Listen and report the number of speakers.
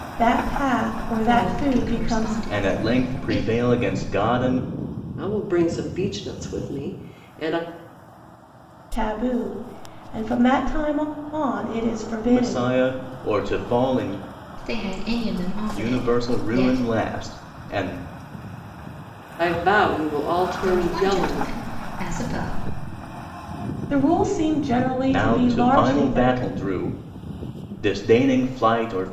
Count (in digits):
4